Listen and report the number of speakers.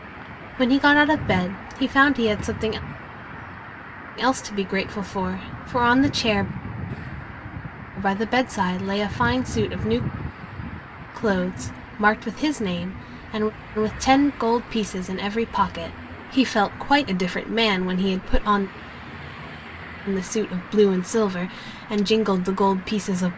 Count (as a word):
one